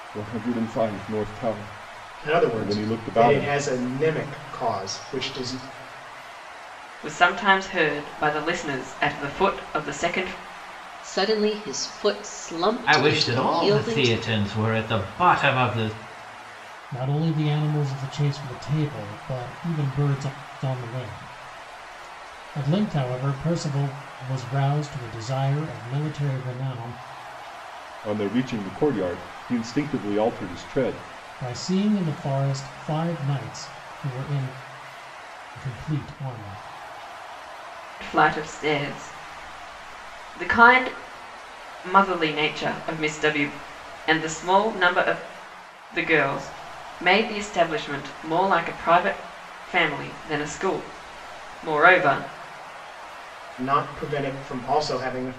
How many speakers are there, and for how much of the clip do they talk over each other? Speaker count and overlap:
six, about 5%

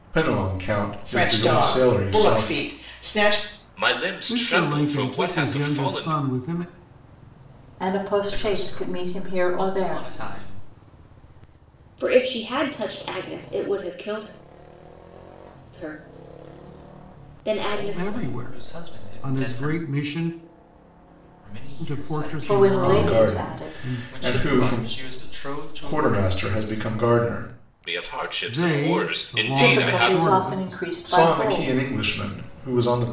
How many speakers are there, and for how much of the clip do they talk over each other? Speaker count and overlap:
seven, about 43%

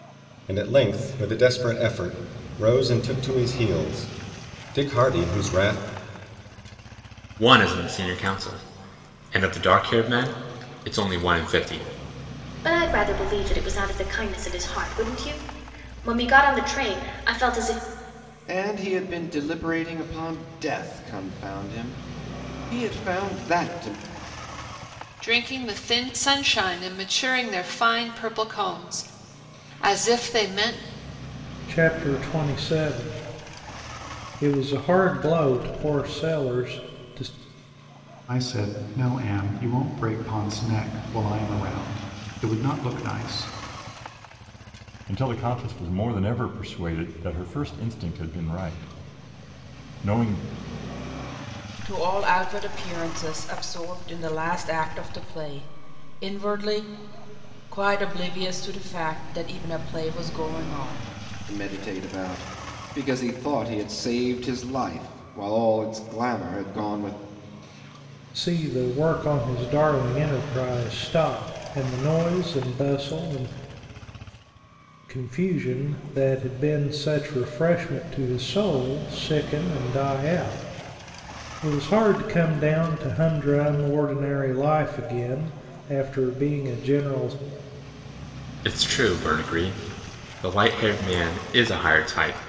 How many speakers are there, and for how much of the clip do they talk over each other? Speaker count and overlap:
nine, no overlap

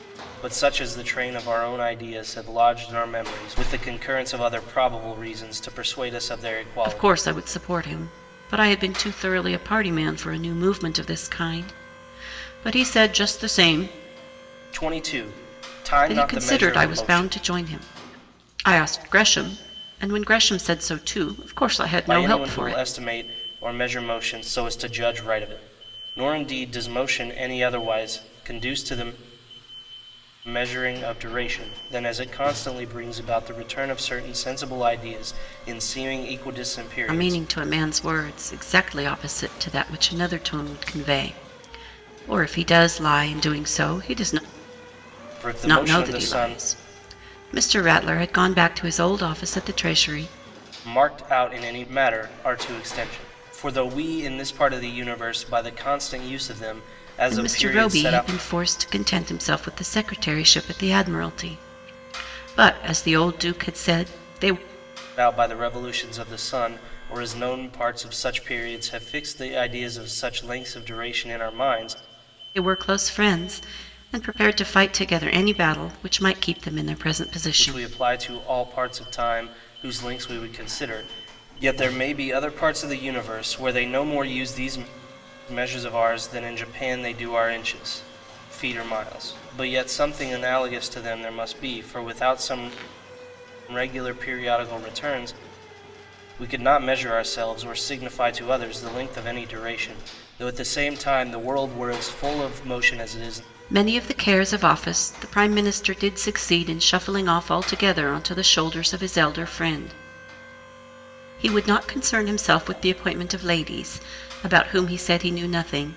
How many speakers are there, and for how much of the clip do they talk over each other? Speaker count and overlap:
two, about 5%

